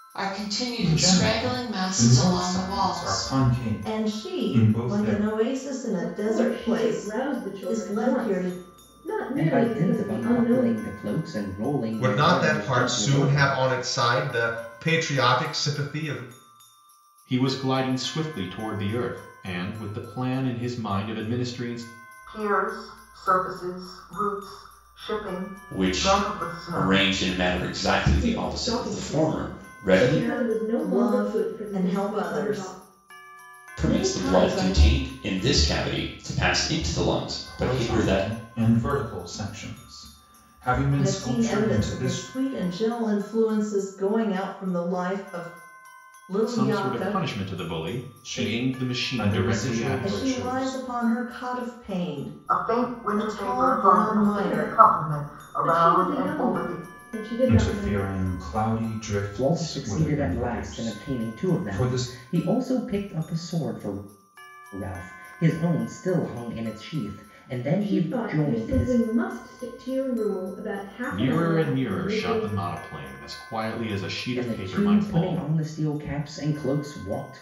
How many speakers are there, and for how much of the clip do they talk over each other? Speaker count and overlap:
9, about 44%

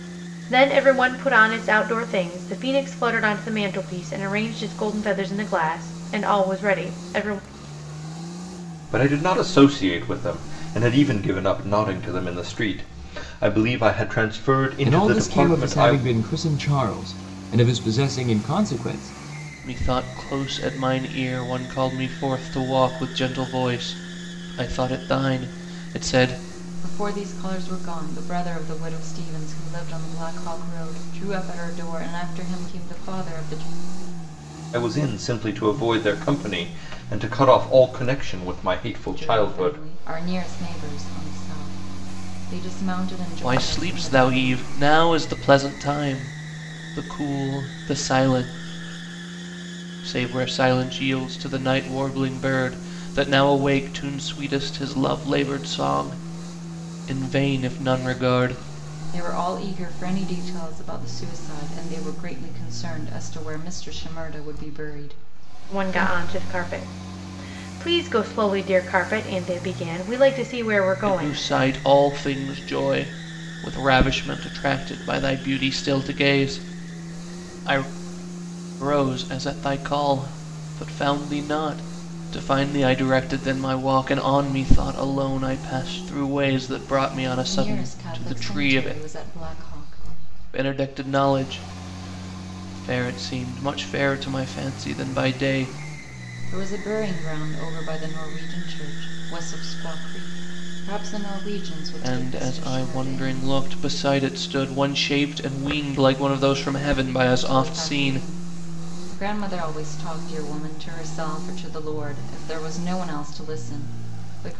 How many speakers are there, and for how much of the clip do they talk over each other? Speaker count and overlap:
5, about 7%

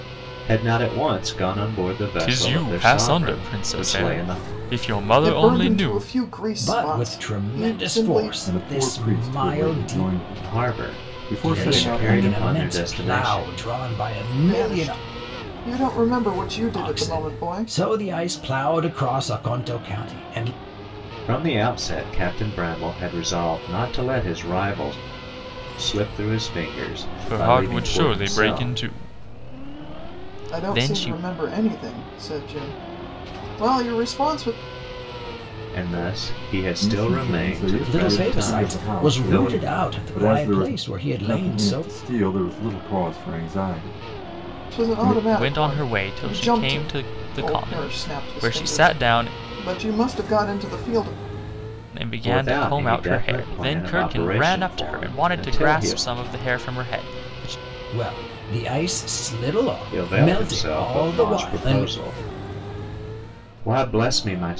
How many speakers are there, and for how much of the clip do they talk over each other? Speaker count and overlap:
5, about 43%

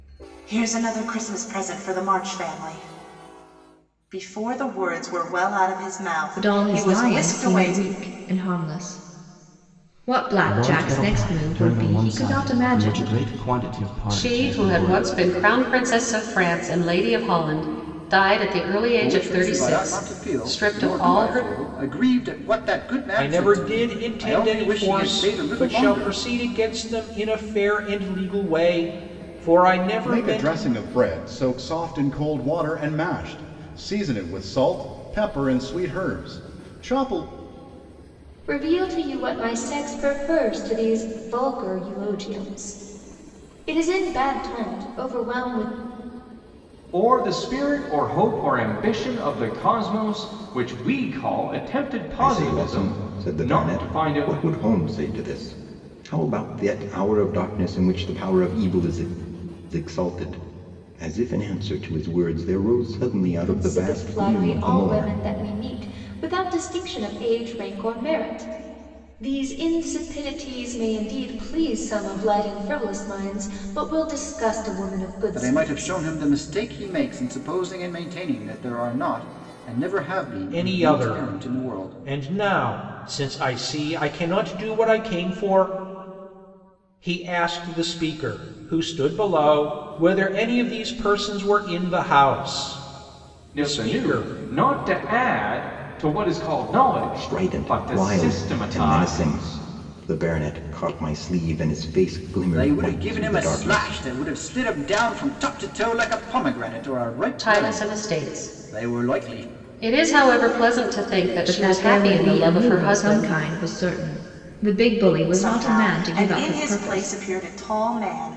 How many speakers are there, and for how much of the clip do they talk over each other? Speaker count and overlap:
10, about 24%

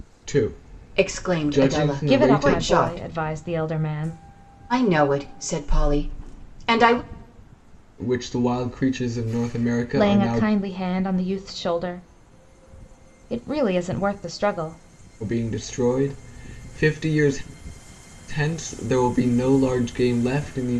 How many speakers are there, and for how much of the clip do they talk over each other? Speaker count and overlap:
3, about 13%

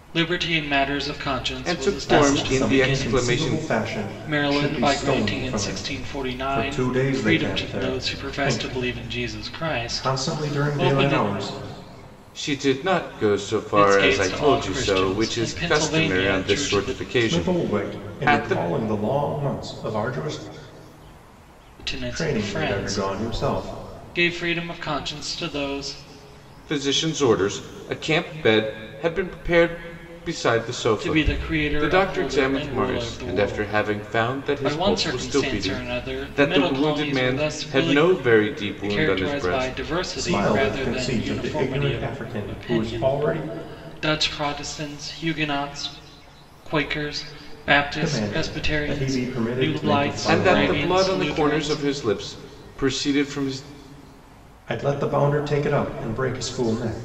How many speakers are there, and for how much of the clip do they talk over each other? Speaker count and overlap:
3, about 49%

